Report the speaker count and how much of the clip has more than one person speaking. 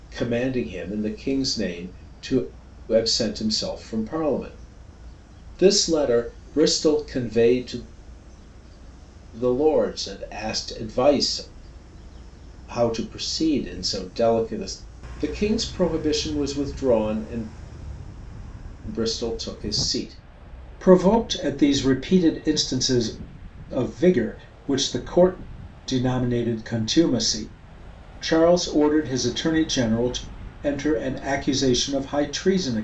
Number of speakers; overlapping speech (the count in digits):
1, no overlap